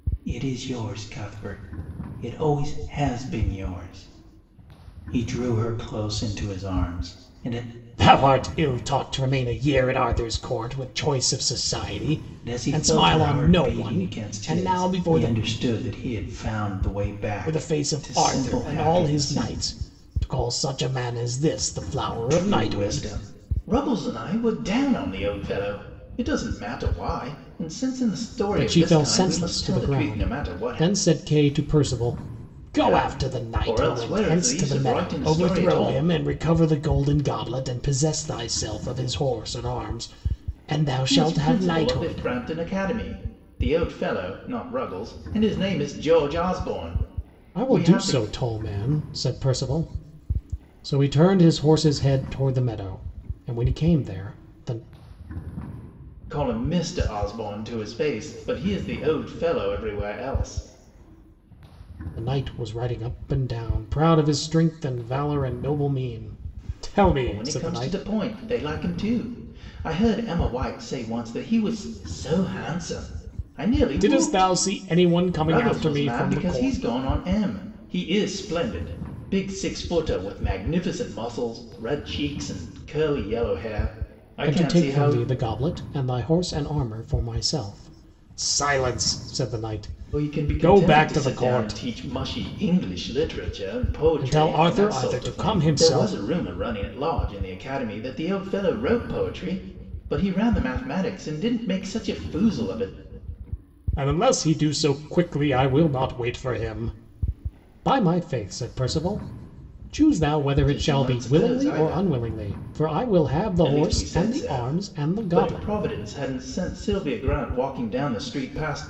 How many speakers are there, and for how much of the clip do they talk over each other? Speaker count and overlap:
2, about 21%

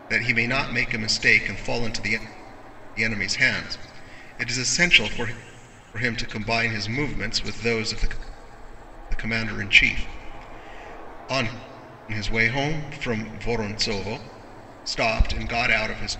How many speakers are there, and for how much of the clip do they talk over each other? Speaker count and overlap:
1, no overlap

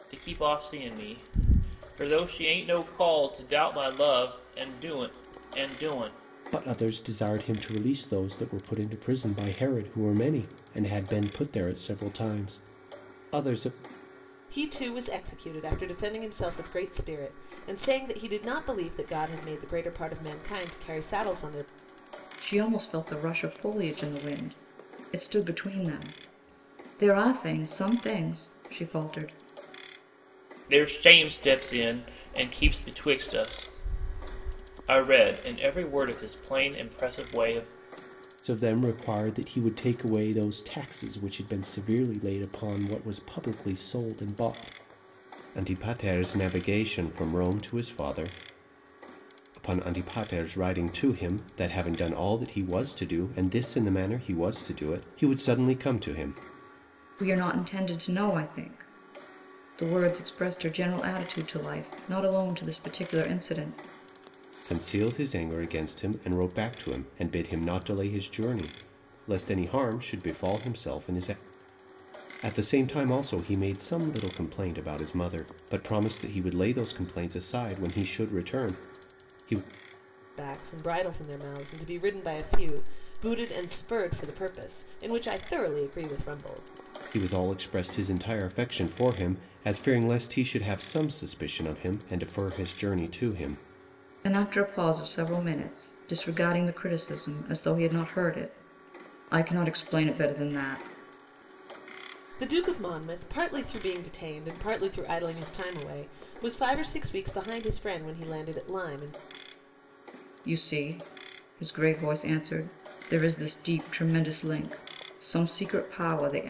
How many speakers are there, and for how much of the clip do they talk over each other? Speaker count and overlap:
4, no overlap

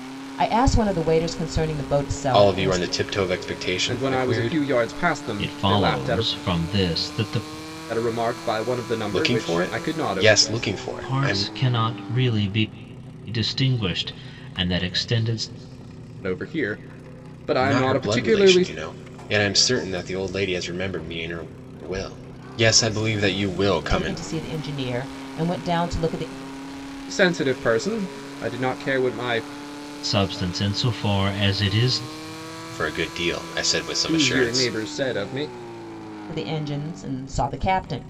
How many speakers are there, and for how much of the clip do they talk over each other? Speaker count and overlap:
4, about 17%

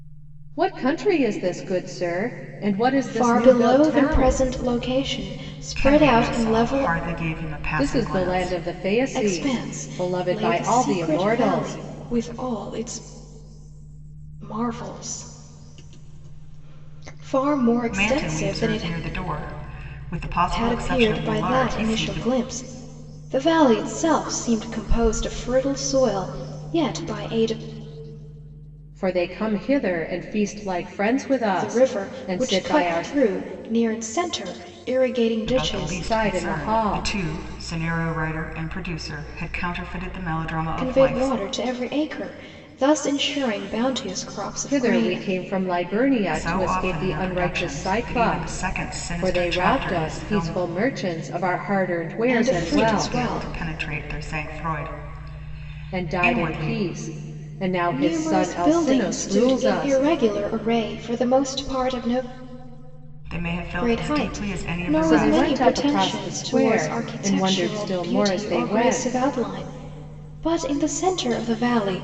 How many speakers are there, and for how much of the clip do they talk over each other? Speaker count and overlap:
3, about 37%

